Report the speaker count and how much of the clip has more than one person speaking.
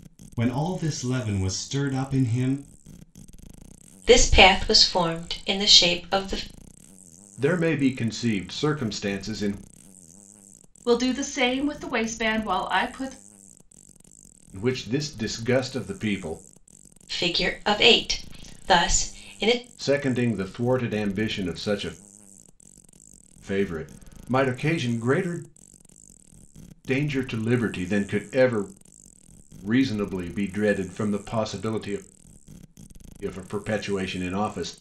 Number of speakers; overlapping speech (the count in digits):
4, no overlap